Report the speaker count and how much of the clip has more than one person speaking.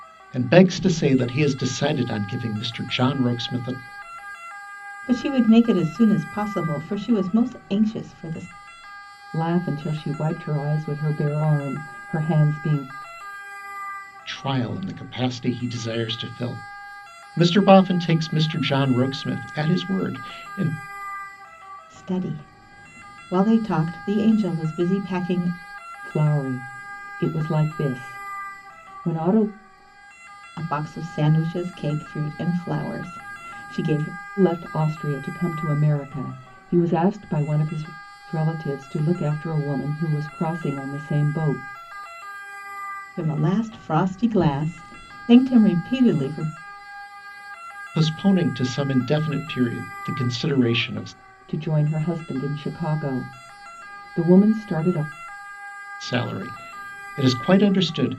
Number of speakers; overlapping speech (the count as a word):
three, no overlap